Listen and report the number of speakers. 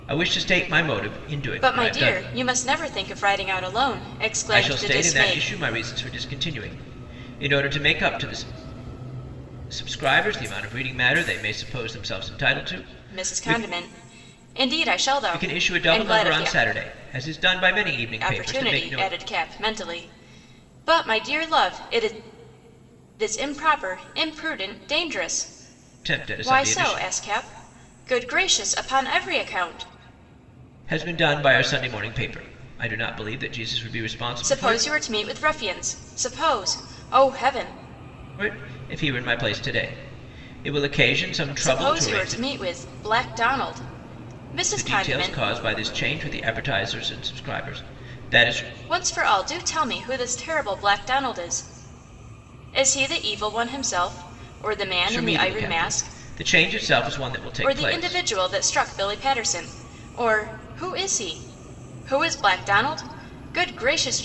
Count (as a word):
two